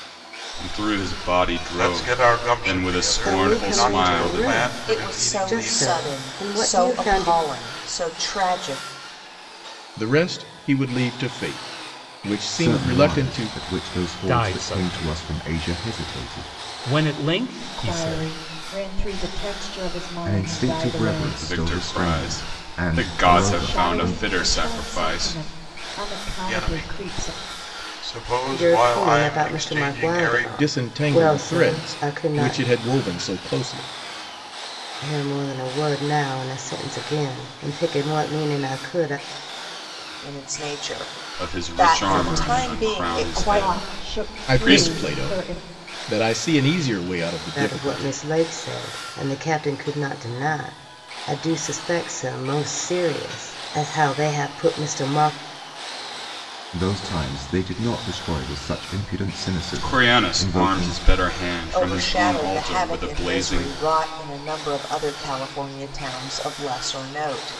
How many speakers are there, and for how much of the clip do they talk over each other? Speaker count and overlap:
8, about 42%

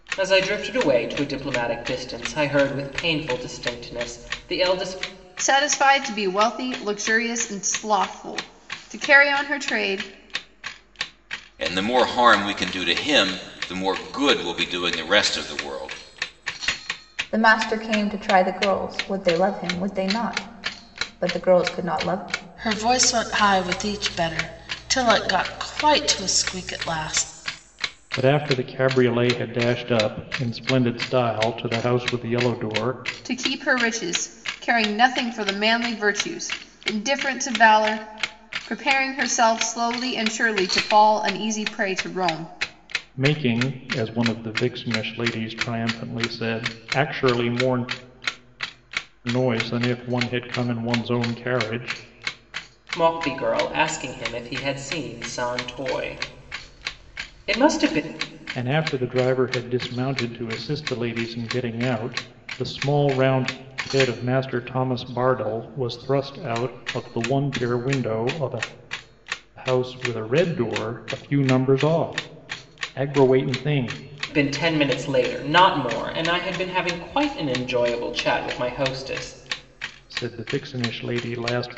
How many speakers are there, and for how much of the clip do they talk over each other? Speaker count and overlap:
6, no overlap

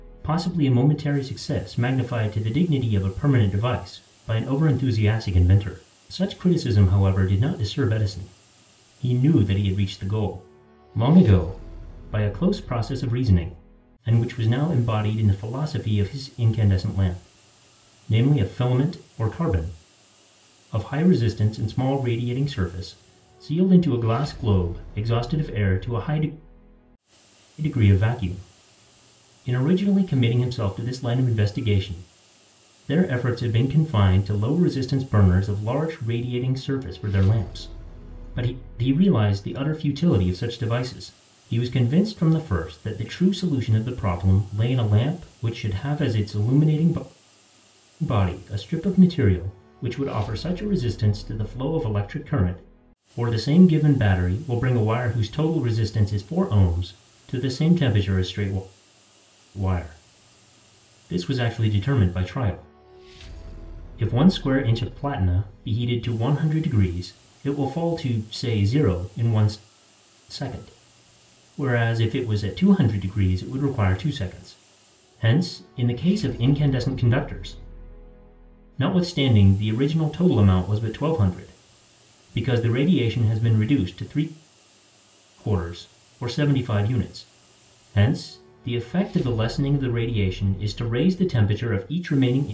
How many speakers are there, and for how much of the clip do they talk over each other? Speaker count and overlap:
1, no overlap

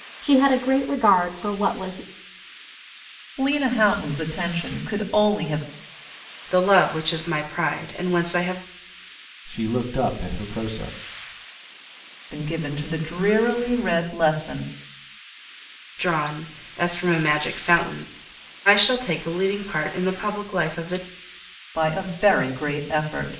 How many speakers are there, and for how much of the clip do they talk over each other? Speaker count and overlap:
4, no overlap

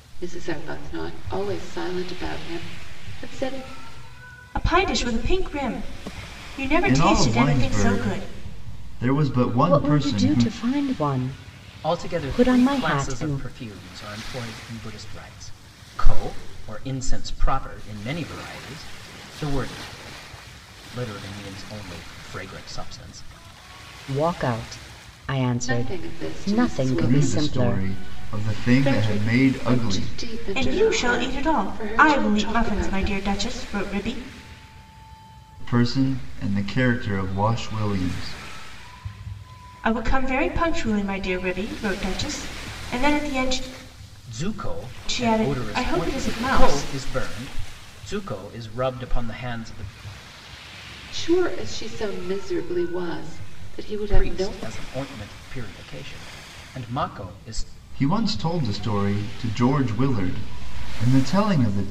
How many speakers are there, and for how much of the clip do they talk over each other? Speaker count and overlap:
5, about 22%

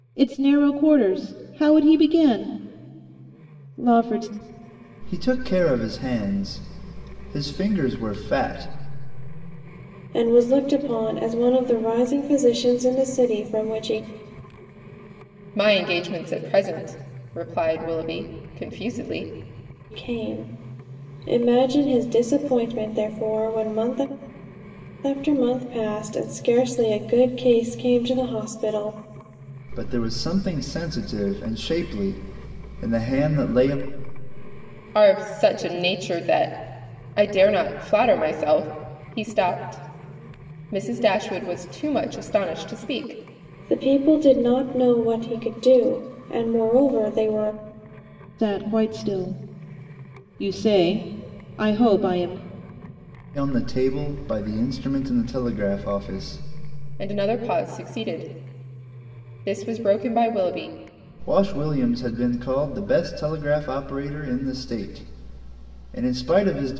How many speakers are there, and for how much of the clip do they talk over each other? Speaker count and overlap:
4, no overlap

